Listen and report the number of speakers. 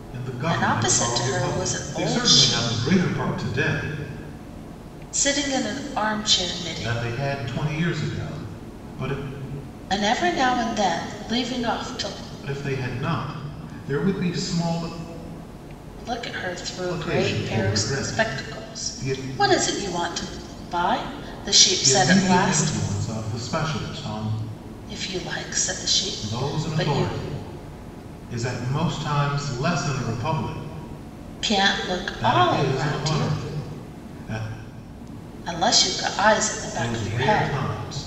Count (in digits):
2